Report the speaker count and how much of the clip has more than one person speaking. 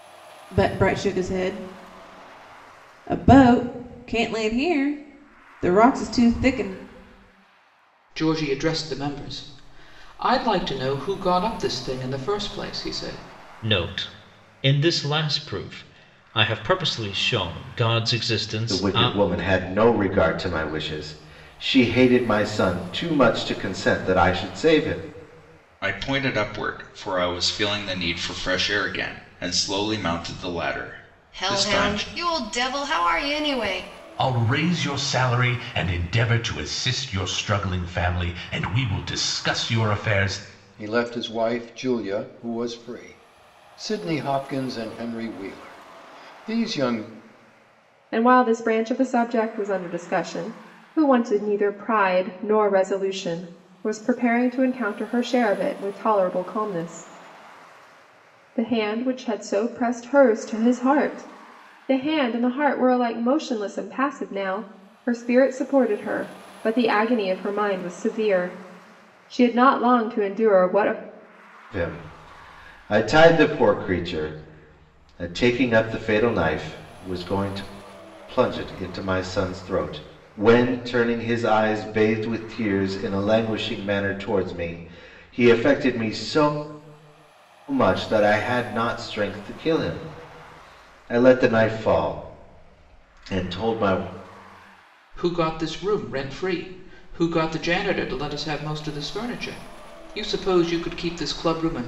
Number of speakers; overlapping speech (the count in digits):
9, about 1%